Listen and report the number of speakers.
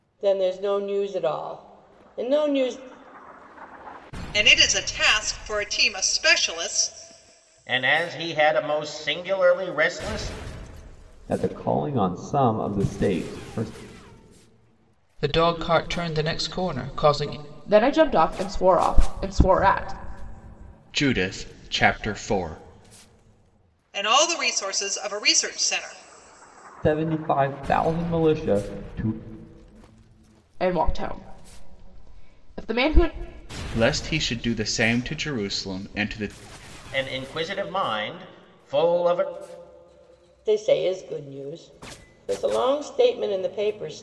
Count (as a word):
seven